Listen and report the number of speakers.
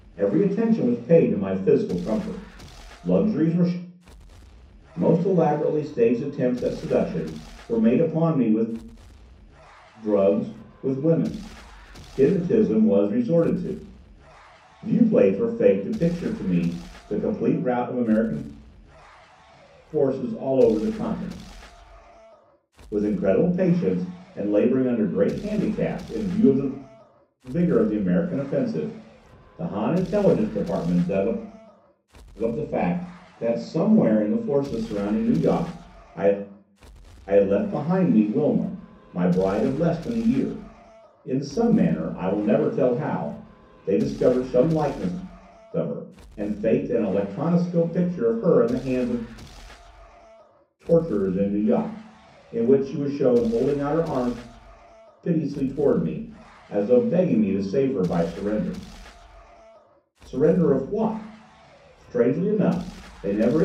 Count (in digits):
1